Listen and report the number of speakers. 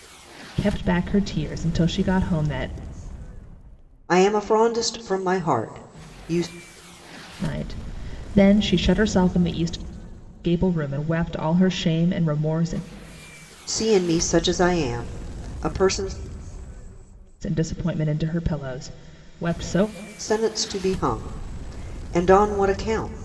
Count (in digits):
2